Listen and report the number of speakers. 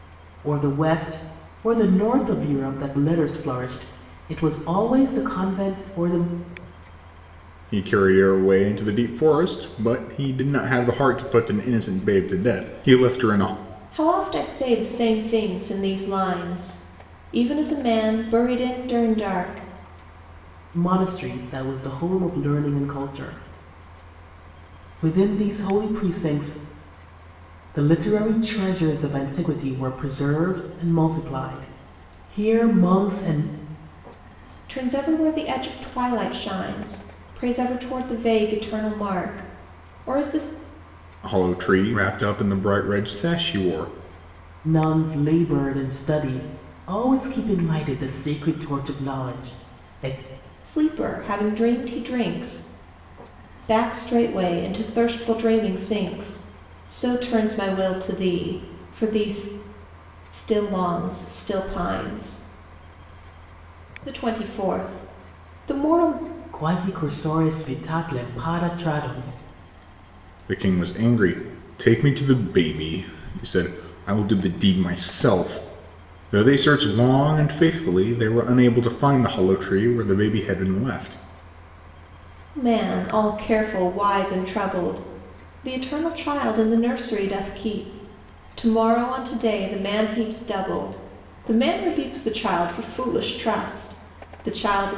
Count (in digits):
3